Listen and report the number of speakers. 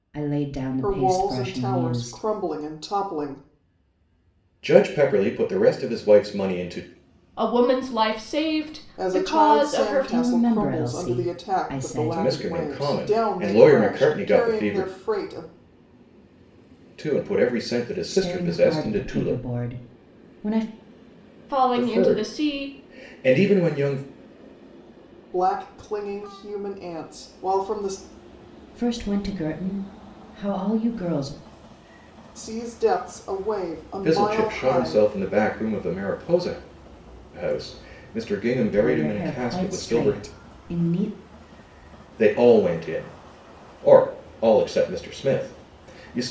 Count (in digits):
4